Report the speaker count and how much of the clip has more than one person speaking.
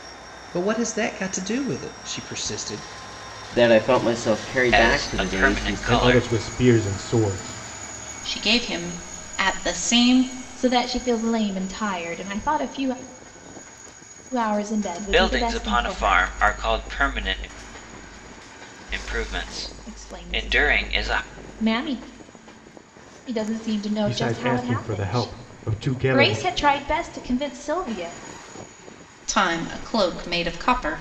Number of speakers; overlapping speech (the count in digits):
6, about 19%